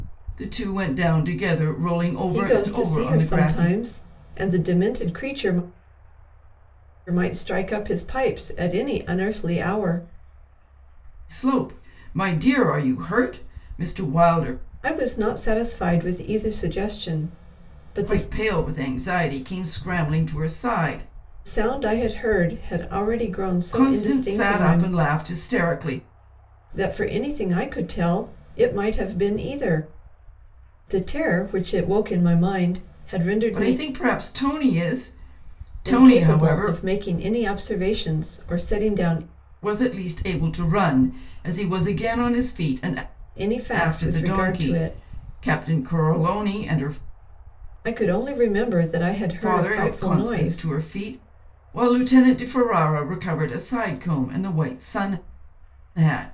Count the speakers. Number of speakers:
two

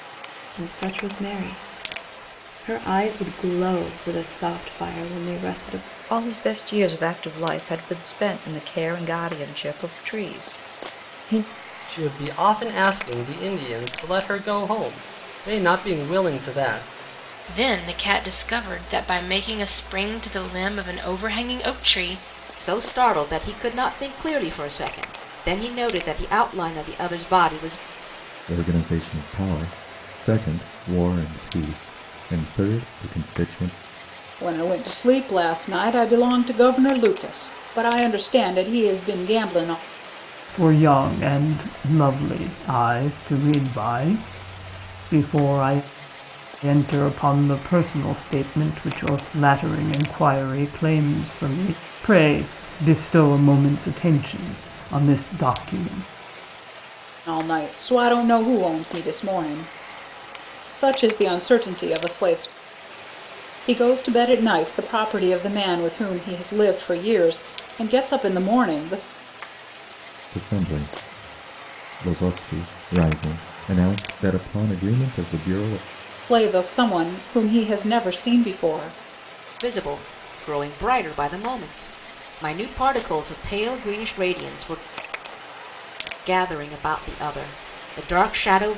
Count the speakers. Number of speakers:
eight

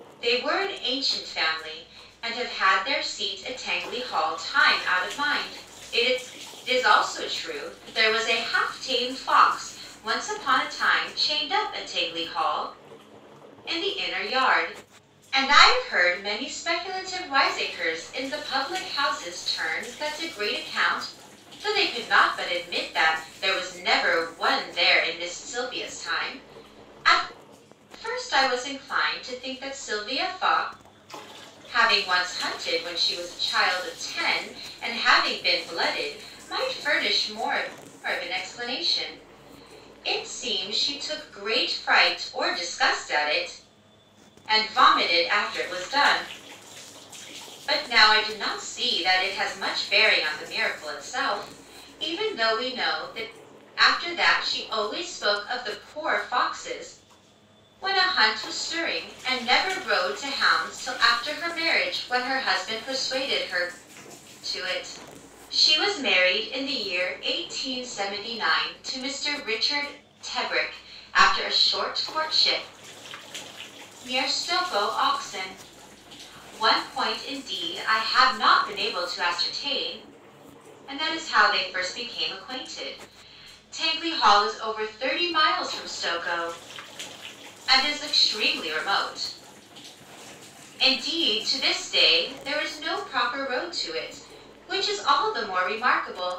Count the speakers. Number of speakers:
one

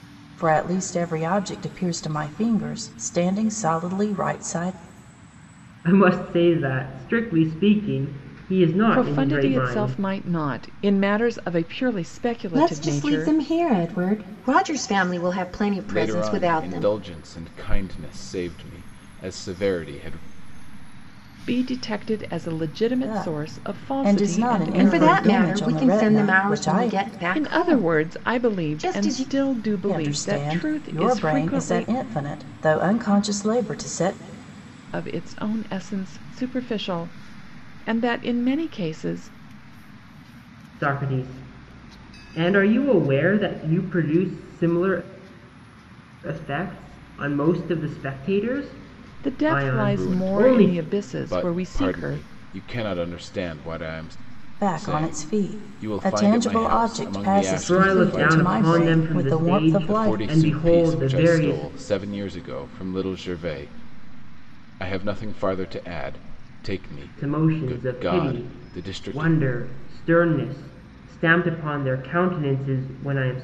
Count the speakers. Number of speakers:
five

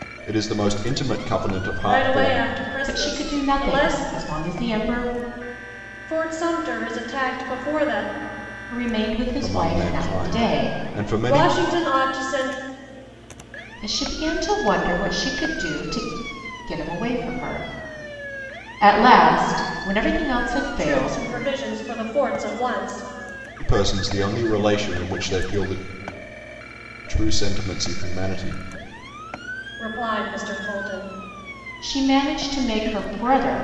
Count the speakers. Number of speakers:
three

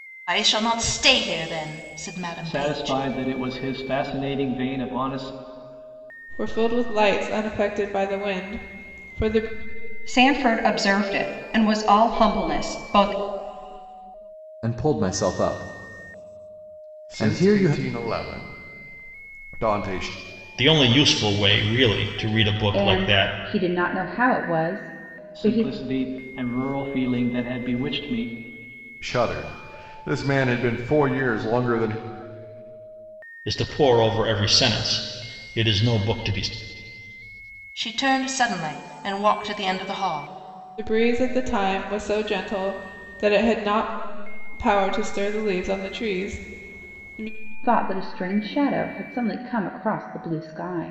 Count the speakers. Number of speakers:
eight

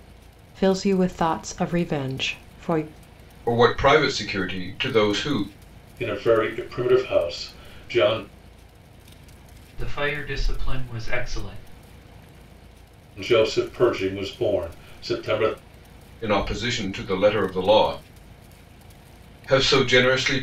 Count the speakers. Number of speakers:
four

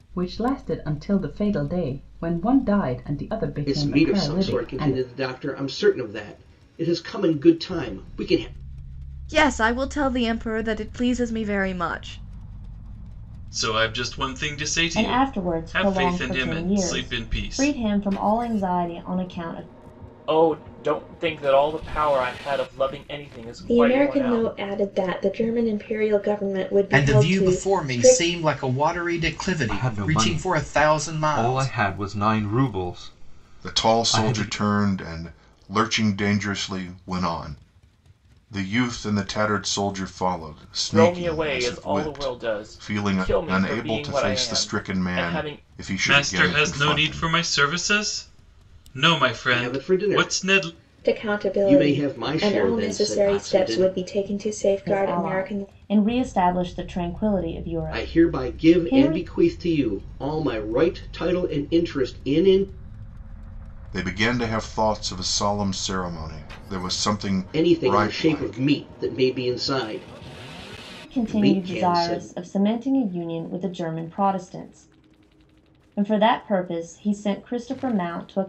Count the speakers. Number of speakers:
ten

